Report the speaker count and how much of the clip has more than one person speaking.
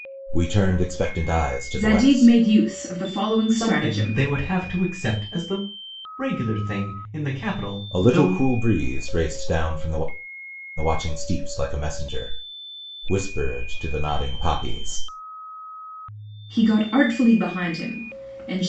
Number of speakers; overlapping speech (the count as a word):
three, about 10%